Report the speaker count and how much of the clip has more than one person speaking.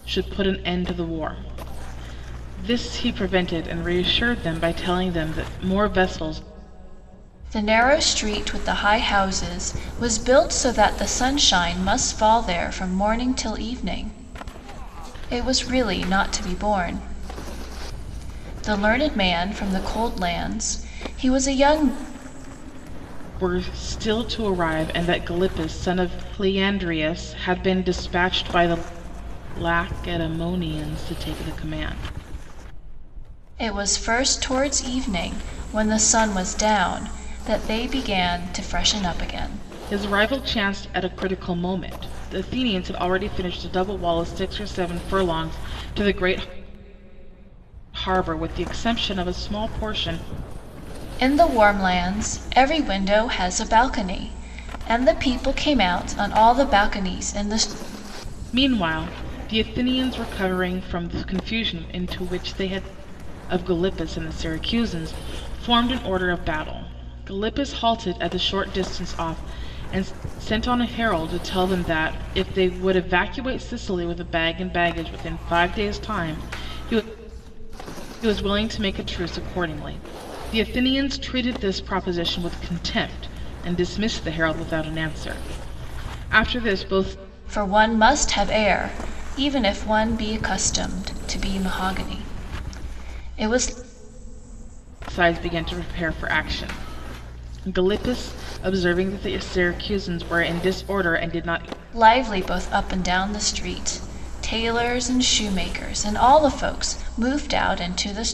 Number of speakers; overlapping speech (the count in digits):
2, no overlap